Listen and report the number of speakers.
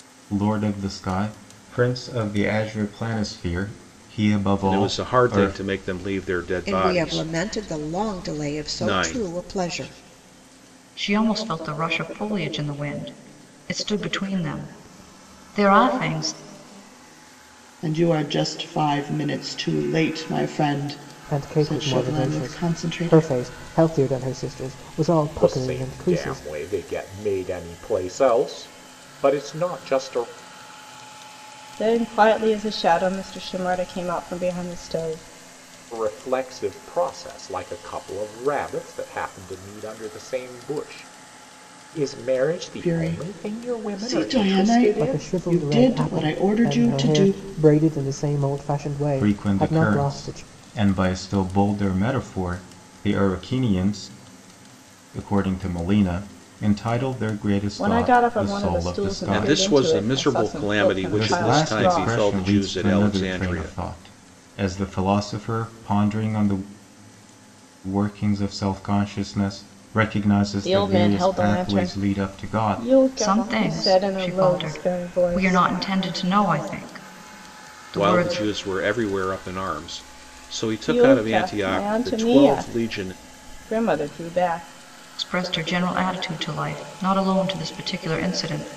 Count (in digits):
8